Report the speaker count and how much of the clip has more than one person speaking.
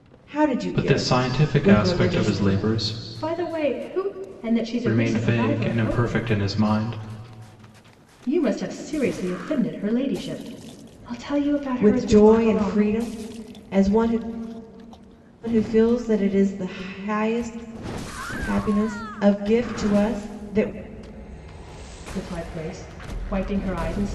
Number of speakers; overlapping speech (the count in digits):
3, about 21%